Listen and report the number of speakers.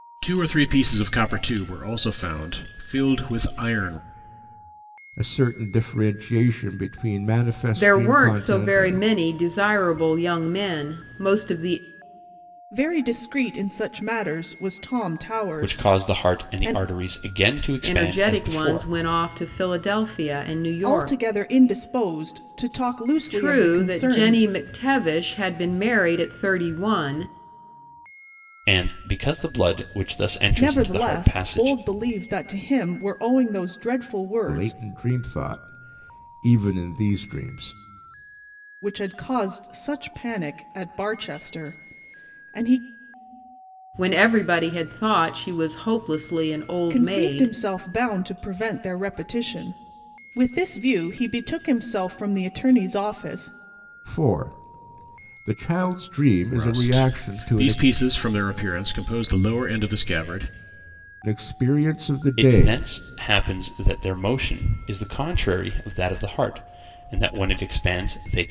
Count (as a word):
five